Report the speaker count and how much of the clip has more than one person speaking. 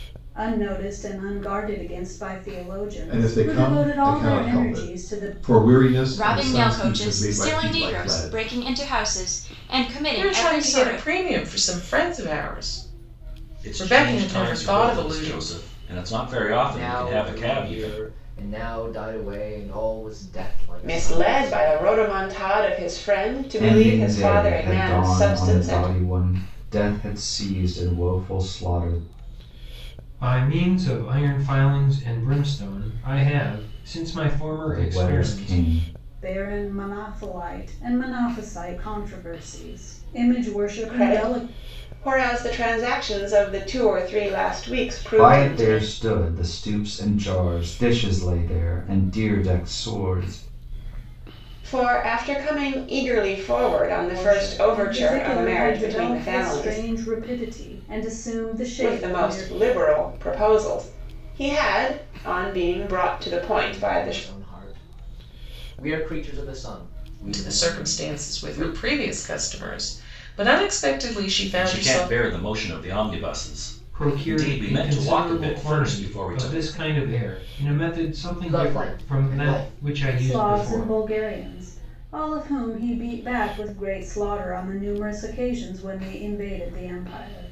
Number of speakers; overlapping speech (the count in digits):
9, about 30%